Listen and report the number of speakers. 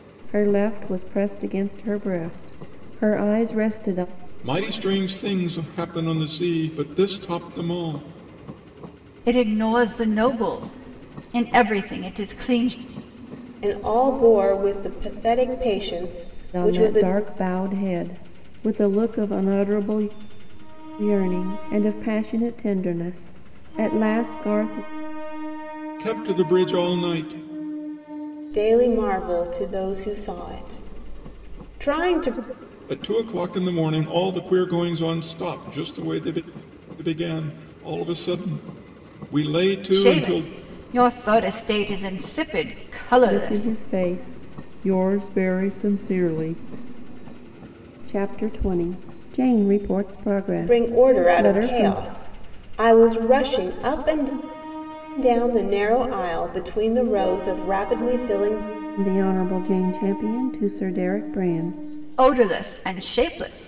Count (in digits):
4